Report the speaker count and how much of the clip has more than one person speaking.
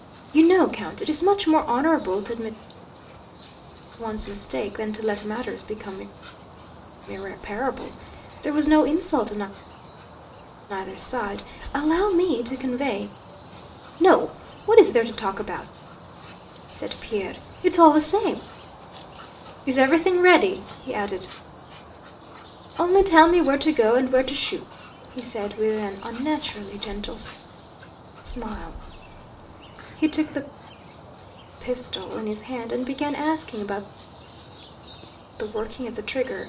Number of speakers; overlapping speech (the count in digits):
1, no overlap